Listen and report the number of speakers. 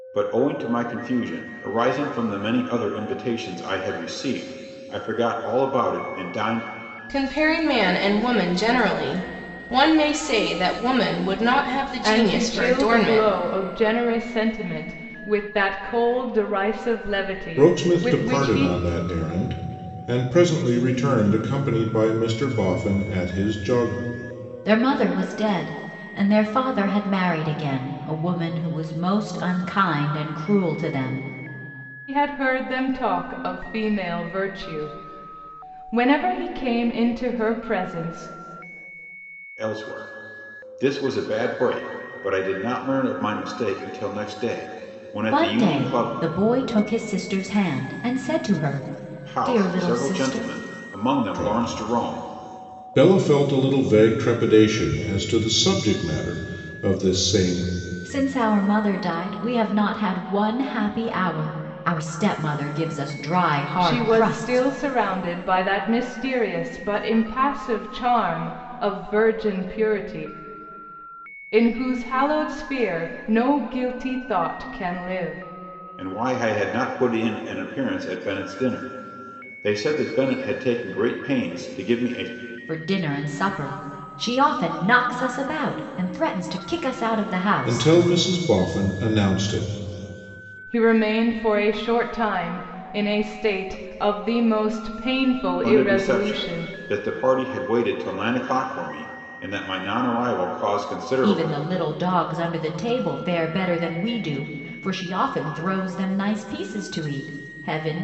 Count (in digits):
5